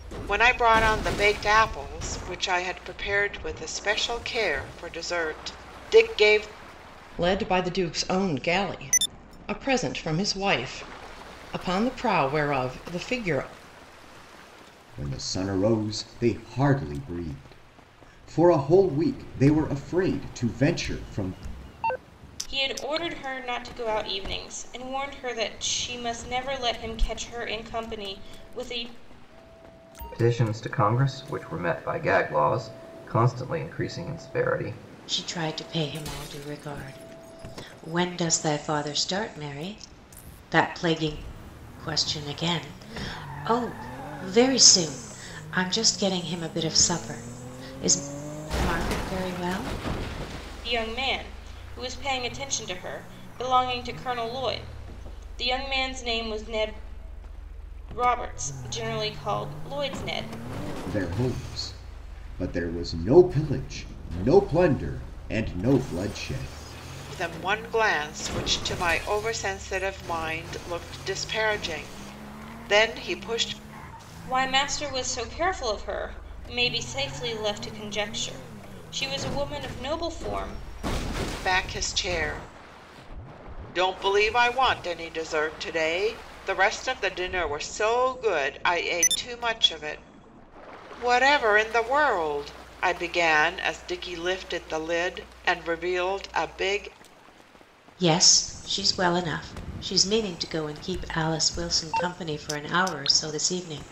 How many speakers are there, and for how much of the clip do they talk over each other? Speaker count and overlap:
six, no overlap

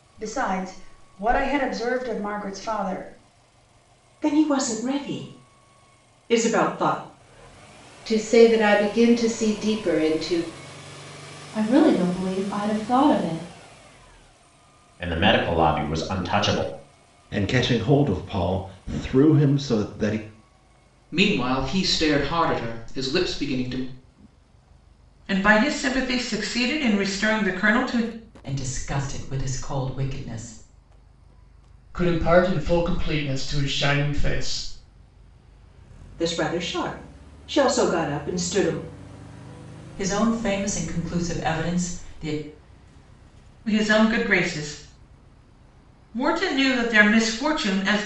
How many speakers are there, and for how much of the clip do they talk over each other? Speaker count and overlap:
ten, no overlap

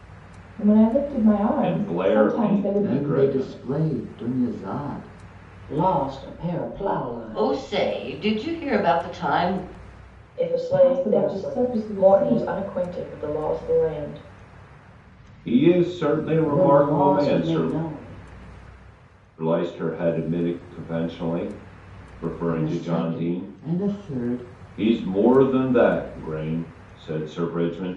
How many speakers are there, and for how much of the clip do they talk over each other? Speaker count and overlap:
six, about 25%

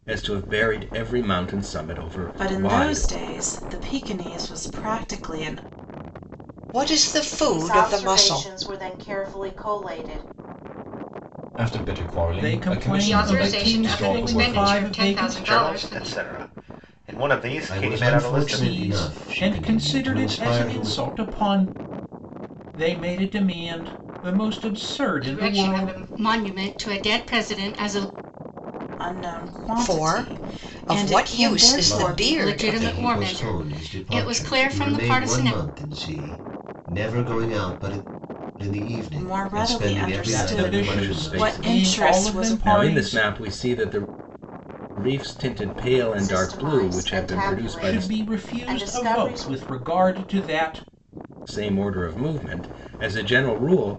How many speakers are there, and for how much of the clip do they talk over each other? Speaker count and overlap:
nine, about 43%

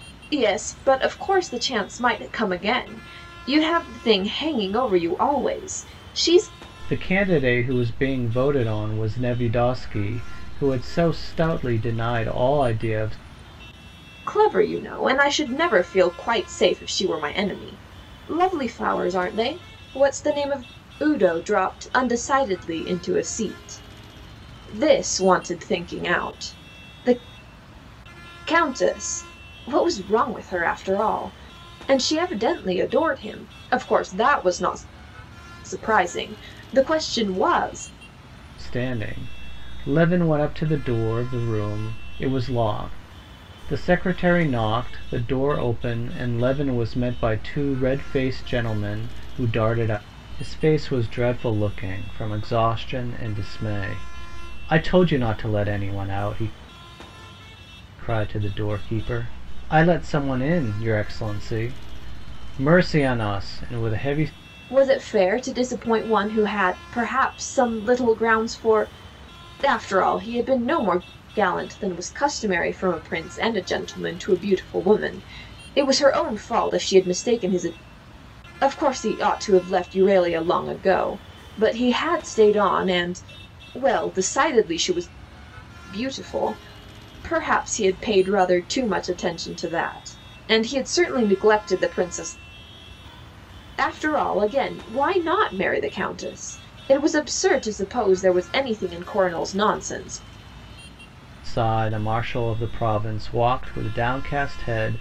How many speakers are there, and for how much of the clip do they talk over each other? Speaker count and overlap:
two, no overlap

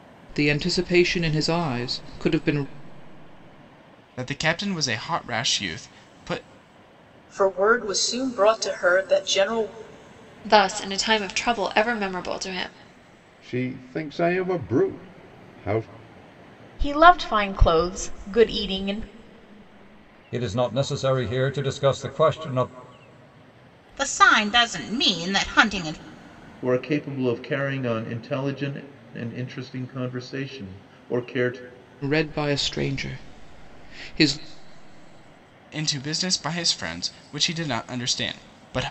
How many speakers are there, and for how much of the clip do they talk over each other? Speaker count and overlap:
nine, no overlap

